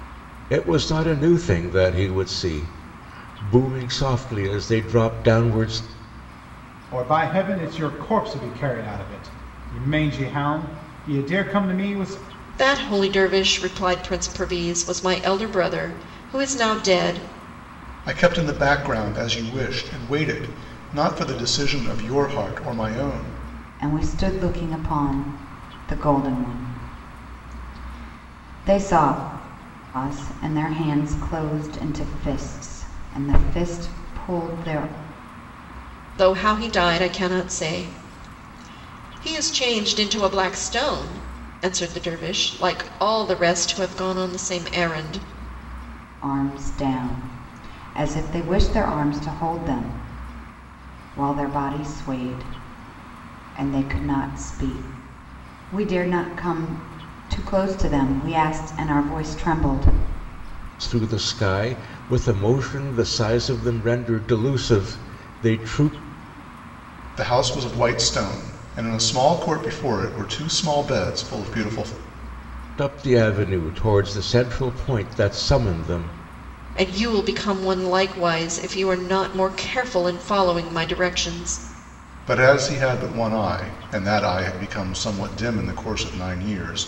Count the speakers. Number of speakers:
5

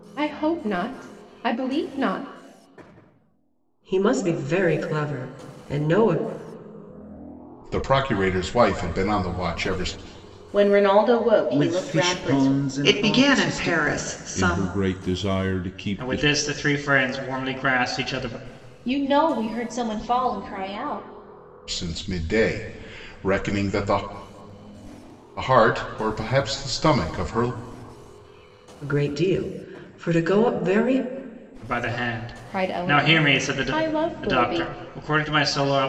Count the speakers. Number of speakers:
9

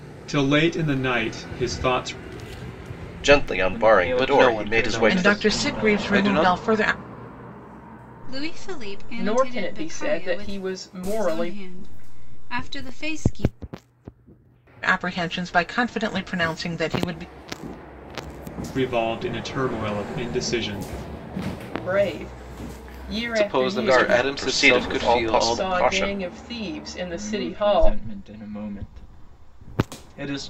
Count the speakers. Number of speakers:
7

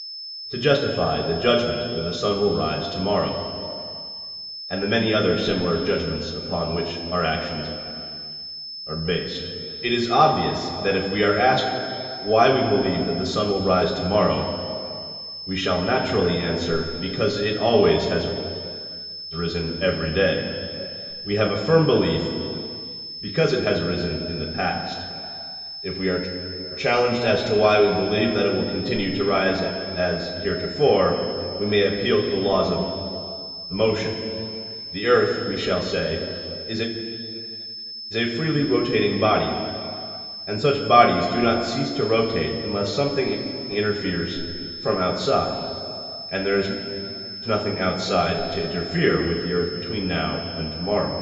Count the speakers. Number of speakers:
1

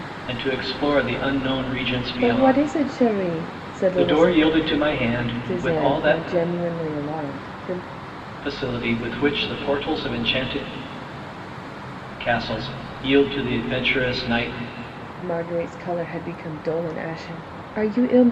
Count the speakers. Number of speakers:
2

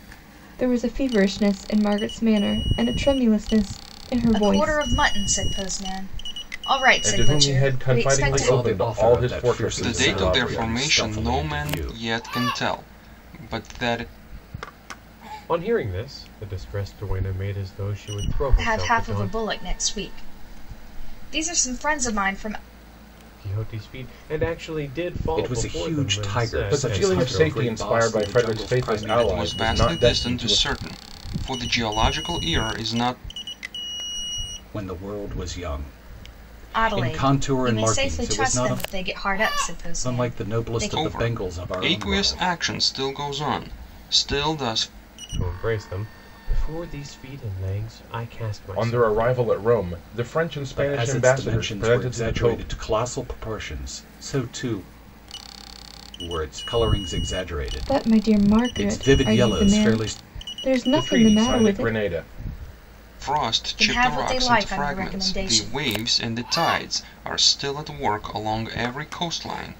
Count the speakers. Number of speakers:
6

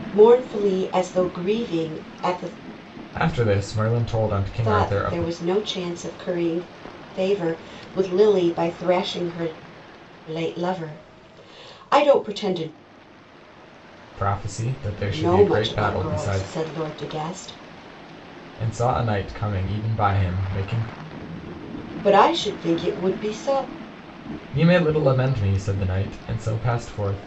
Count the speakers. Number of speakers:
2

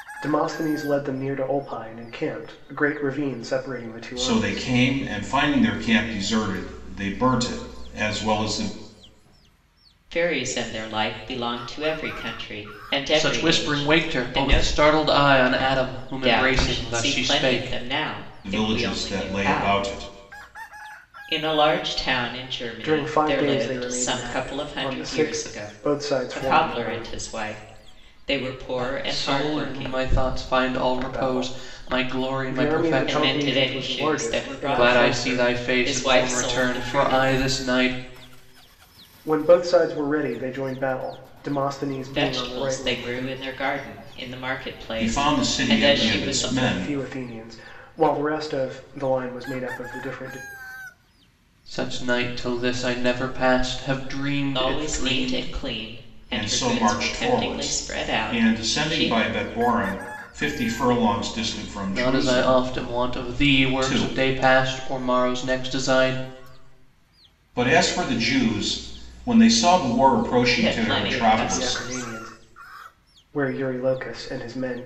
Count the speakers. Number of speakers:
4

